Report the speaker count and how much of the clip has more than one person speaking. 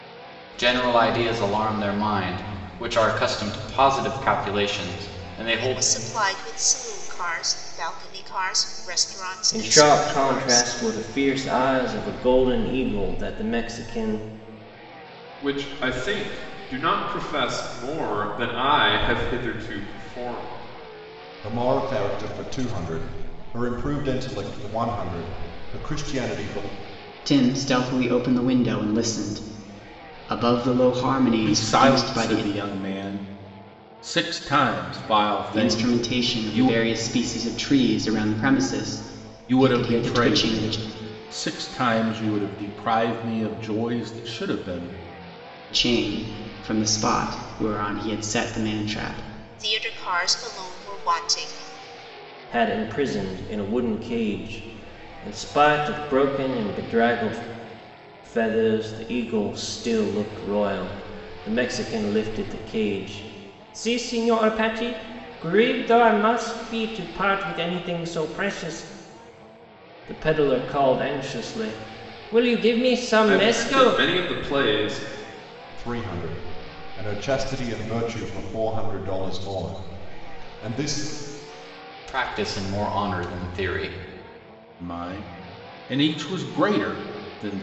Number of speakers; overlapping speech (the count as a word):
seven, about 7%